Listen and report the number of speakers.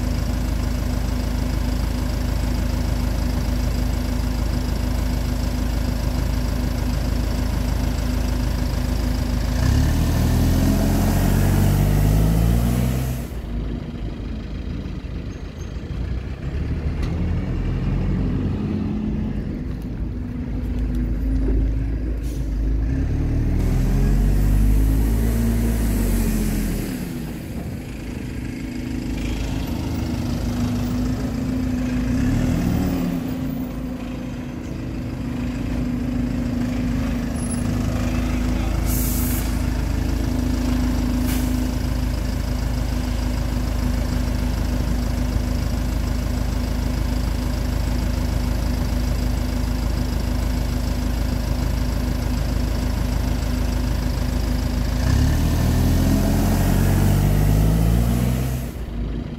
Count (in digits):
0